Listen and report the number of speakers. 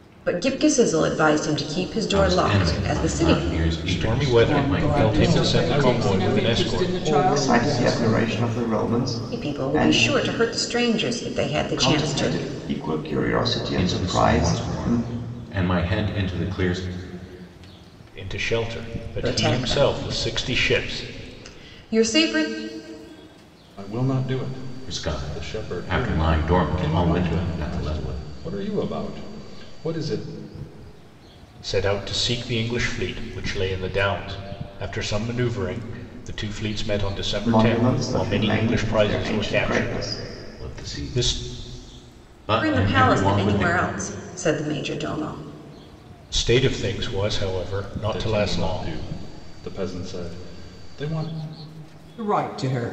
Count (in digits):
6